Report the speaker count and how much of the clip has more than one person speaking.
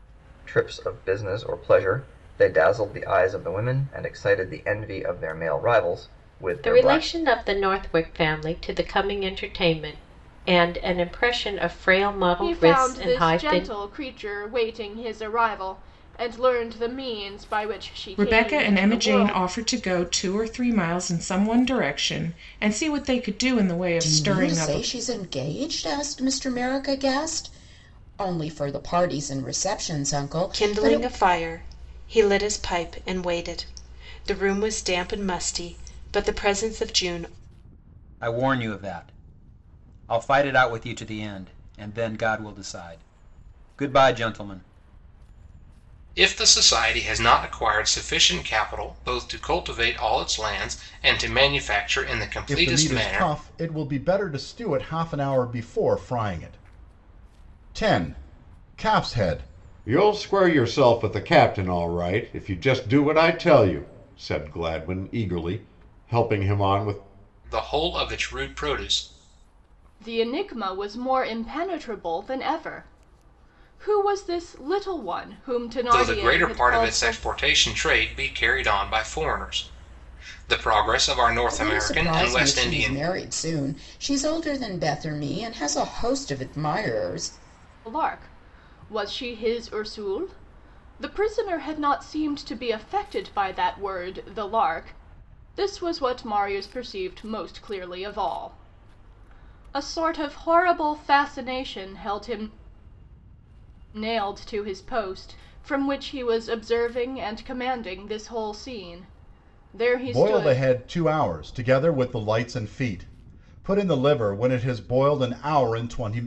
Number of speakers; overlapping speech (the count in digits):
10, about 8%